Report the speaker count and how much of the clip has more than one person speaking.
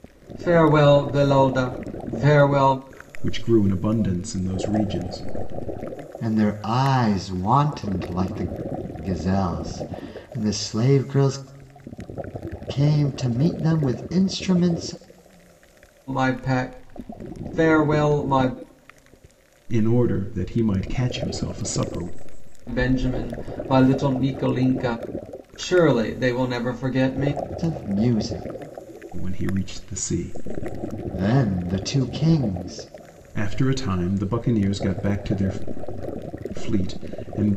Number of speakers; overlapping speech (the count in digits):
3, no overlap